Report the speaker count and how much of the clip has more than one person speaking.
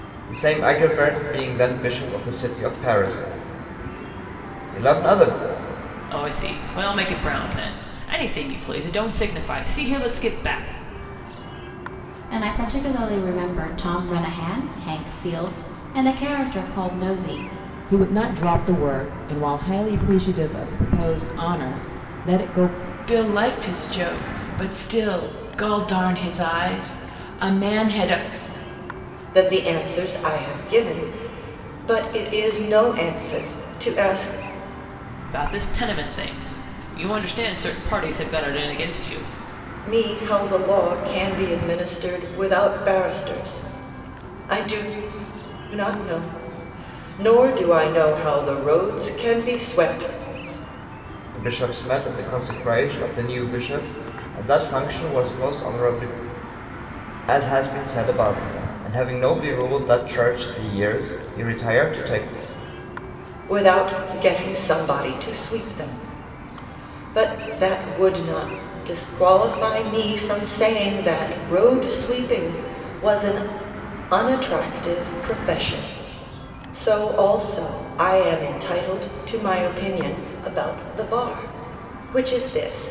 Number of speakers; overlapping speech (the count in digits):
6, no overlap